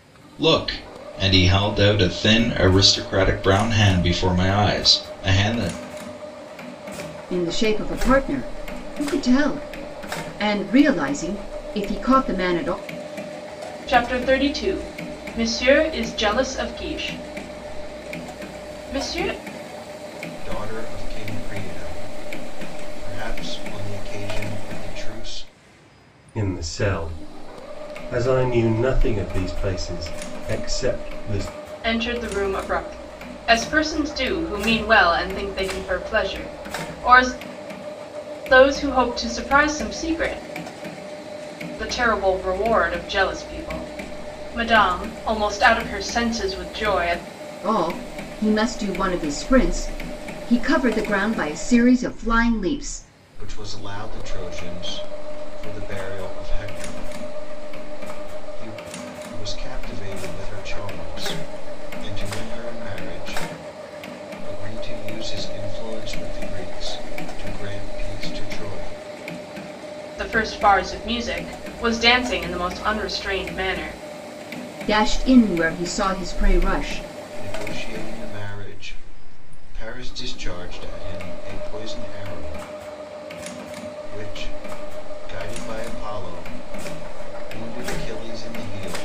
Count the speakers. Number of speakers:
five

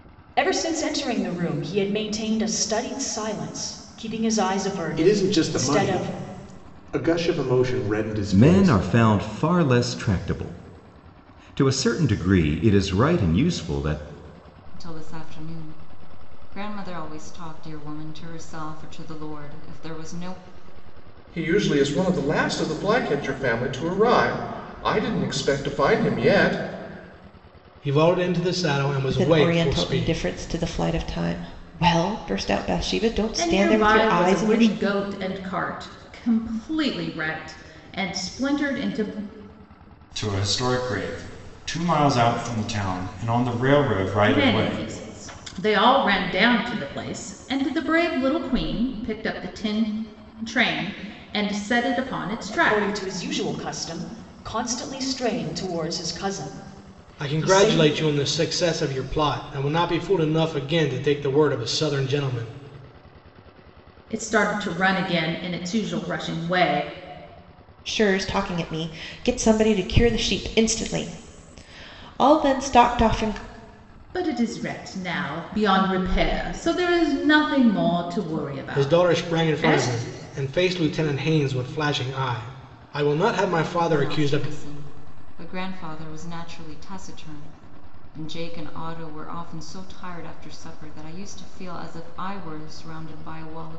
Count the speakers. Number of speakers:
nine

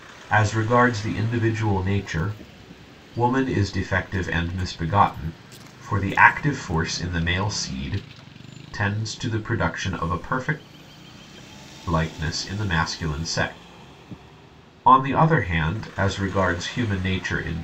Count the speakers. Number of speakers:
one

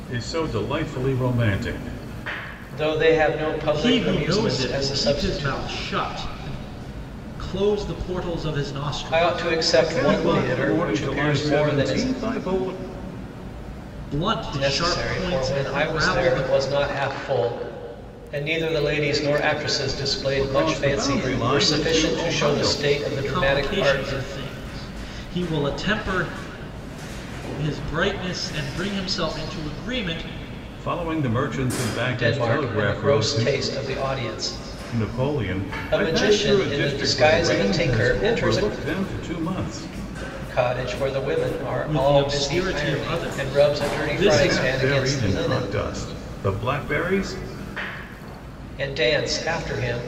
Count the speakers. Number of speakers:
three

